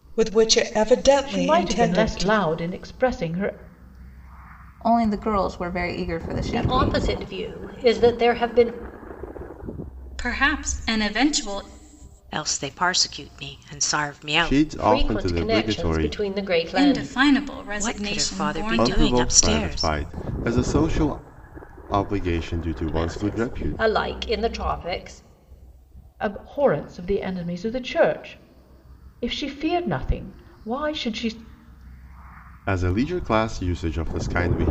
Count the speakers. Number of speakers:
7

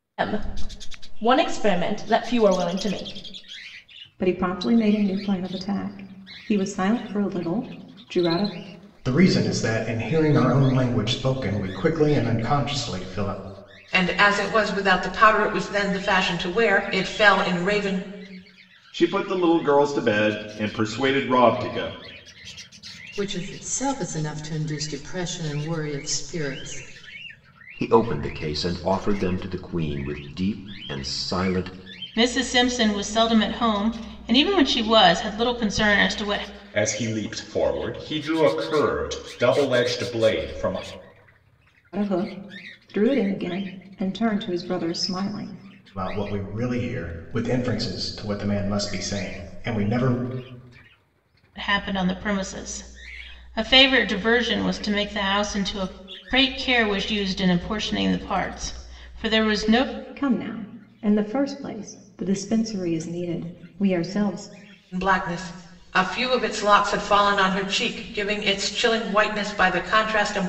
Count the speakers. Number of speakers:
9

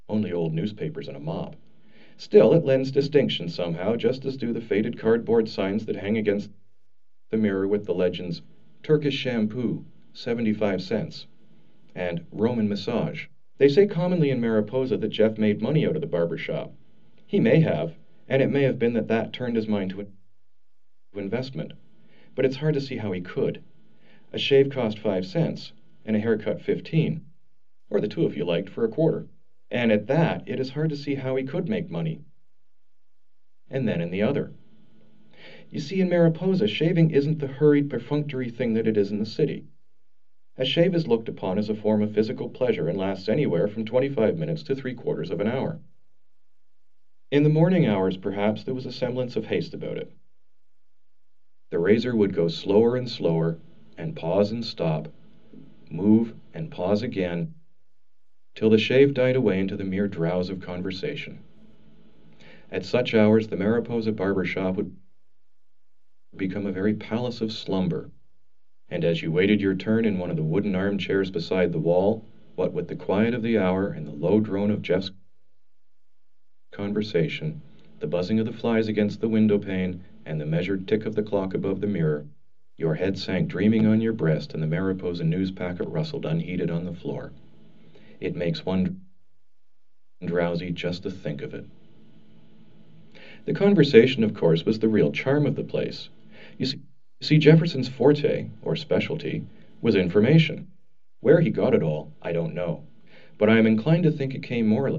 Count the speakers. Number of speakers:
1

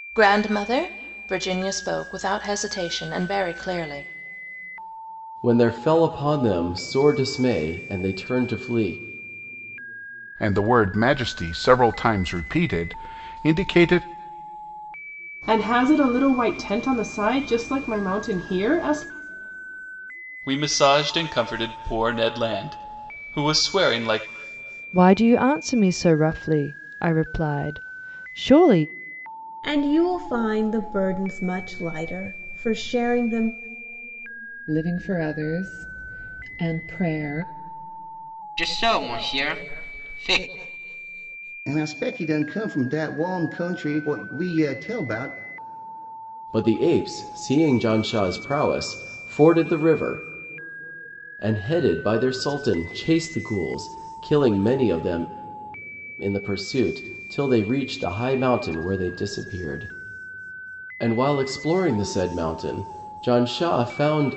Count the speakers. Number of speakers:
10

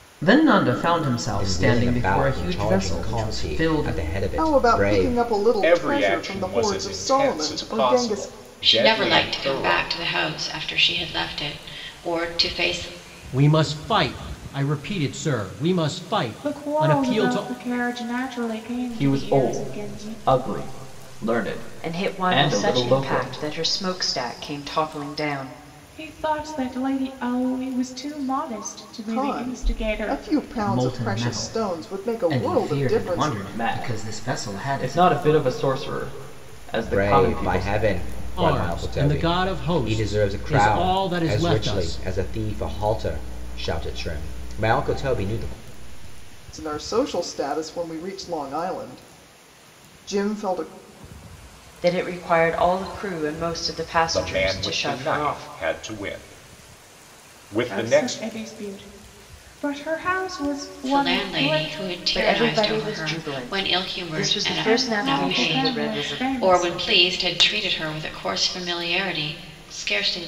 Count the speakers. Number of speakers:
9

